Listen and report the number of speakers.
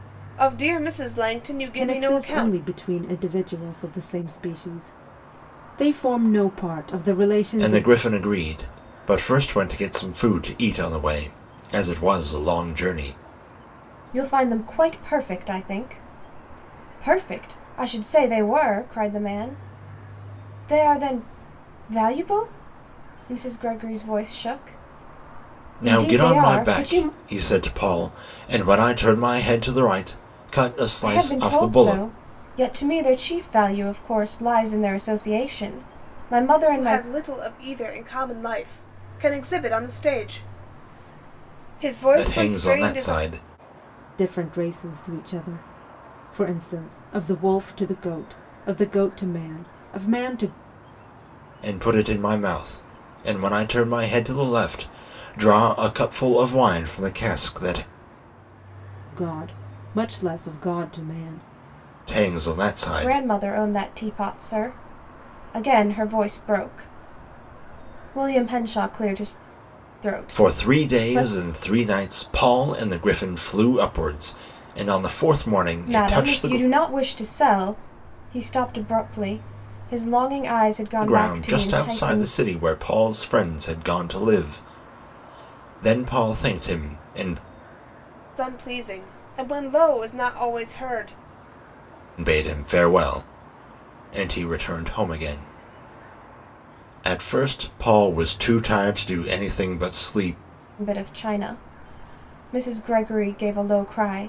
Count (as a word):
four